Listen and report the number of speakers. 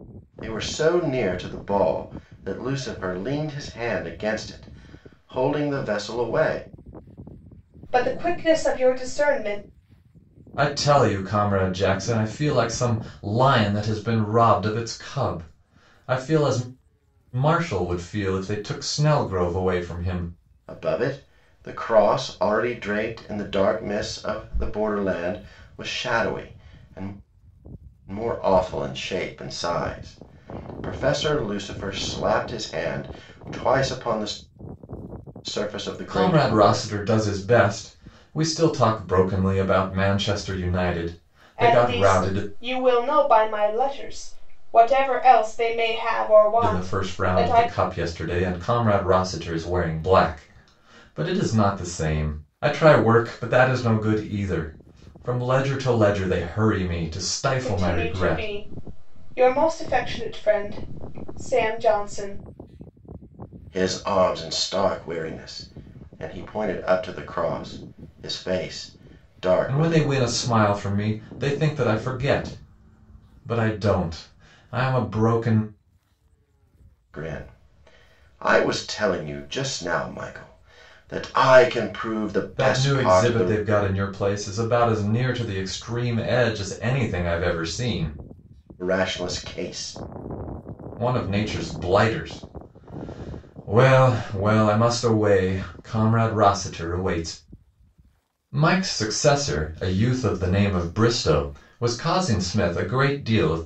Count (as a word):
three